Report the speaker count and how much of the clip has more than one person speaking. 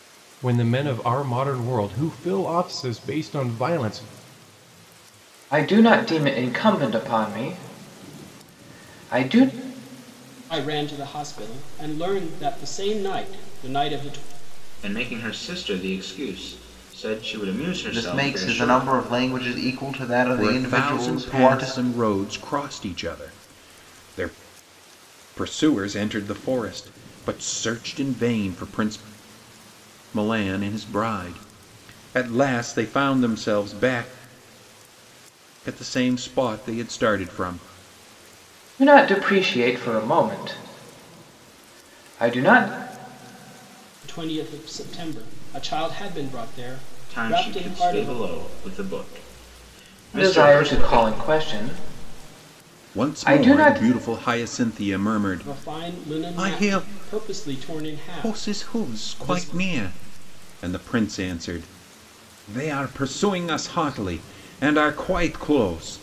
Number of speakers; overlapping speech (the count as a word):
six, about 12%